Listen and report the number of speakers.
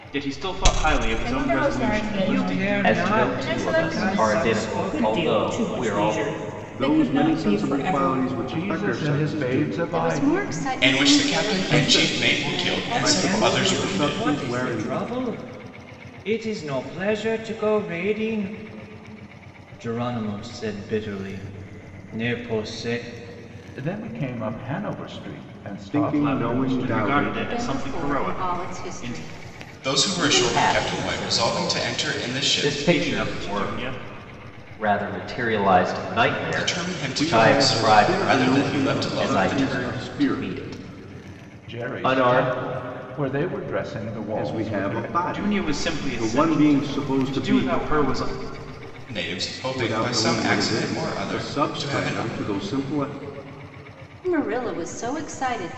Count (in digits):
9